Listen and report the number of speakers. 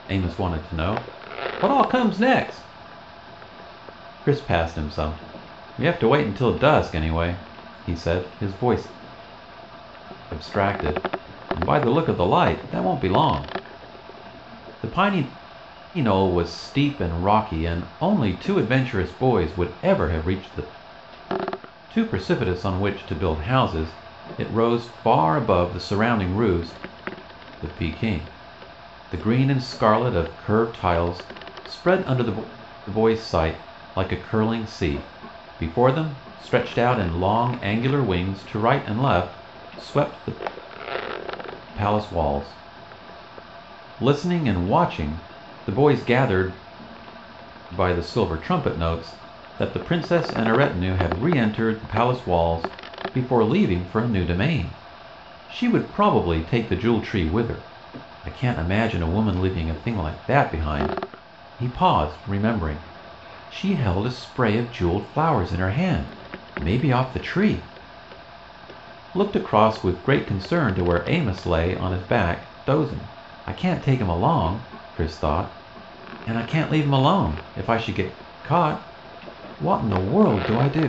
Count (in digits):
1